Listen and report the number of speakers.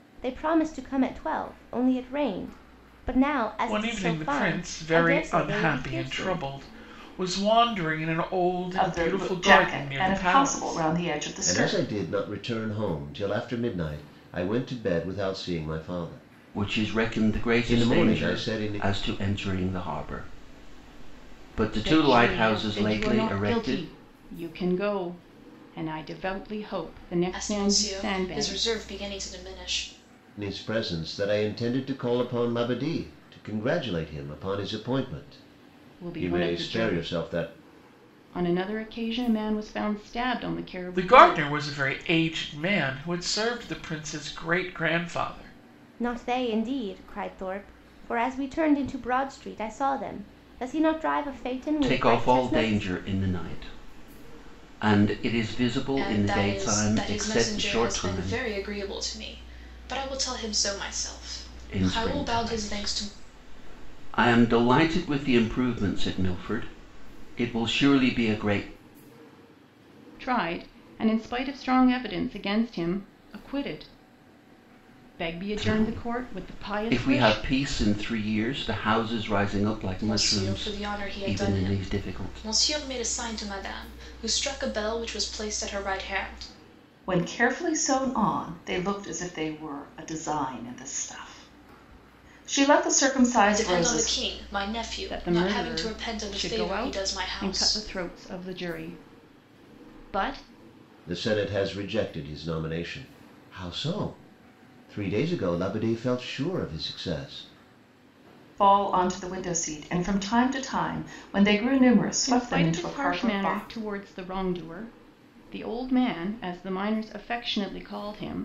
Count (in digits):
7